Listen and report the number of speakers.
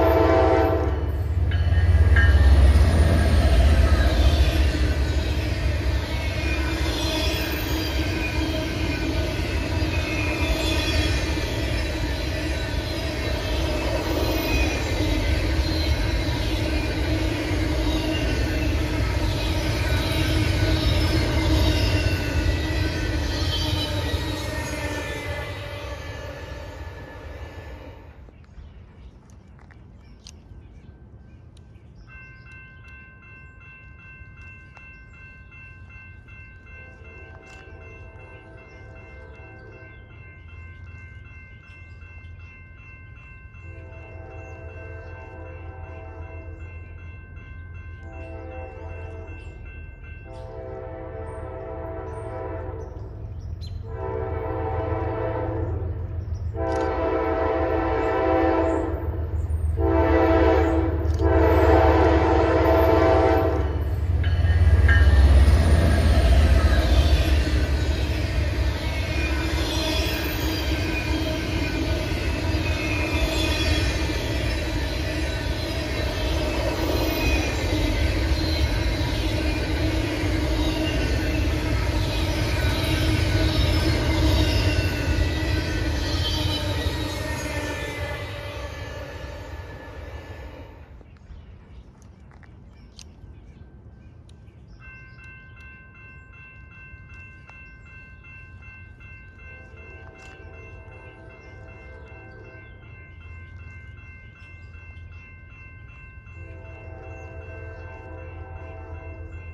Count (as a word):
zero